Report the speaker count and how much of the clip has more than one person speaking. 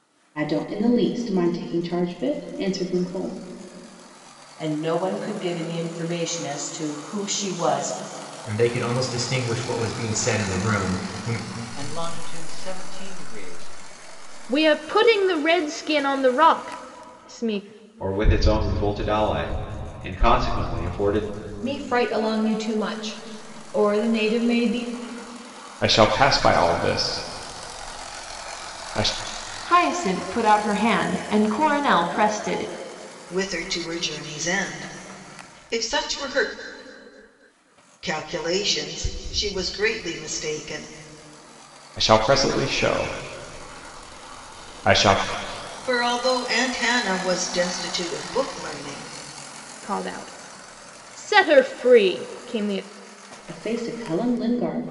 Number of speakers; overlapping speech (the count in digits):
10, no overlap